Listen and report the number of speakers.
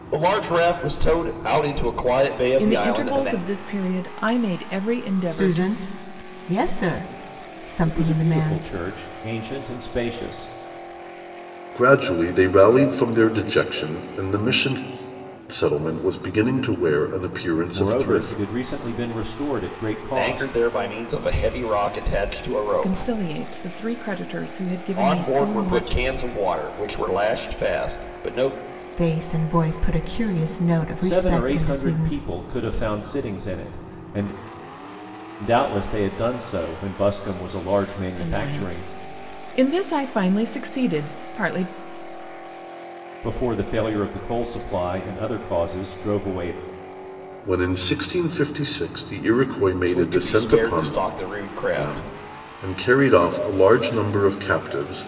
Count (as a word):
five